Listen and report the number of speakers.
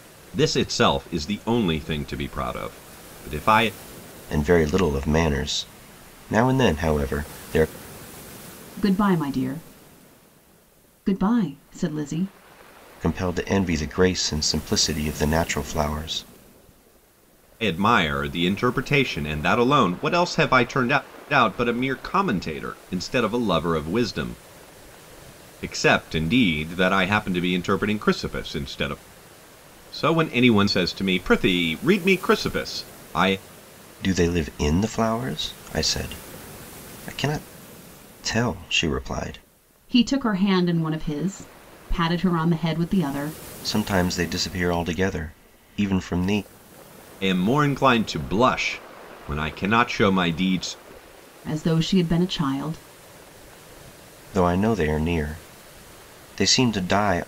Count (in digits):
3